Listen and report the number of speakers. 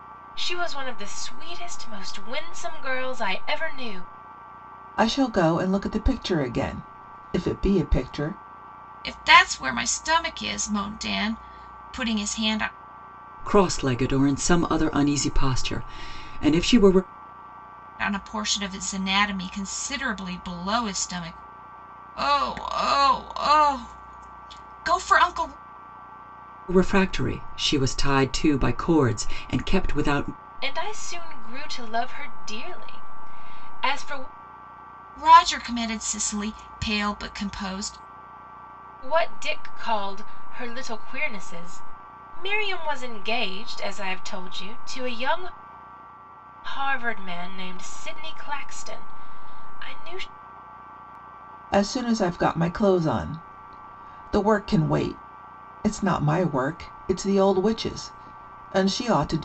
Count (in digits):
4